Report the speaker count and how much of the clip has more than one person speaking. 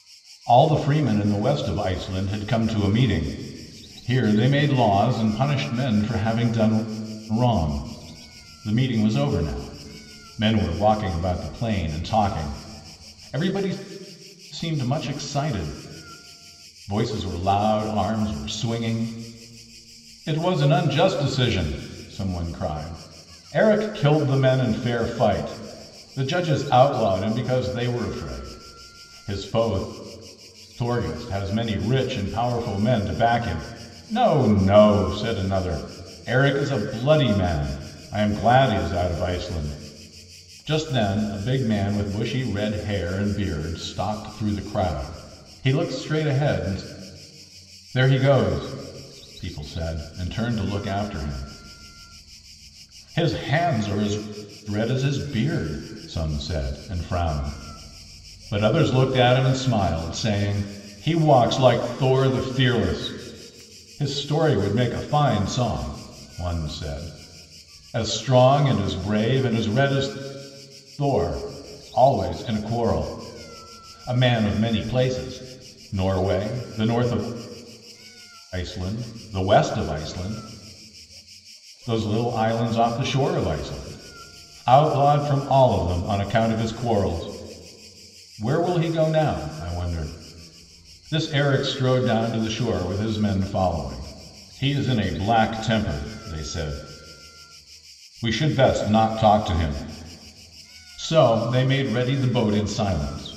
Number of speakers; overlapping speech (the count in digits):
1, no overlap